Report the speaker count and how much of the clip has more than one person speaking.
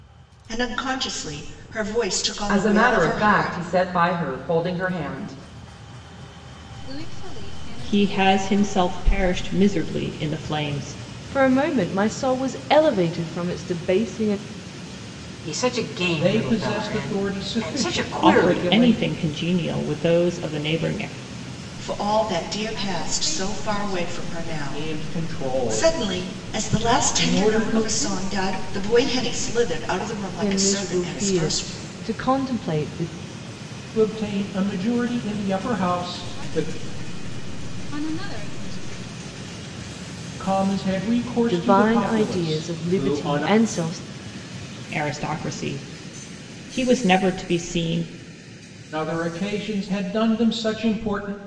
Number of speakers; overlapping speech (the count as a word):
seven, about 34%